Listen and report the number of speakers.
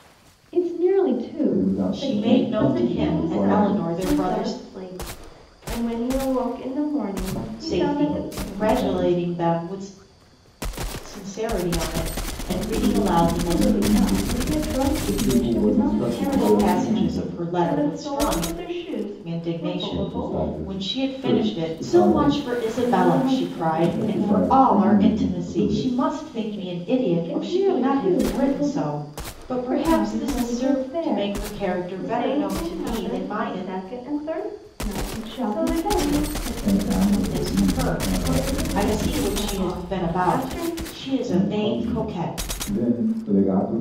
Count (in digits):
4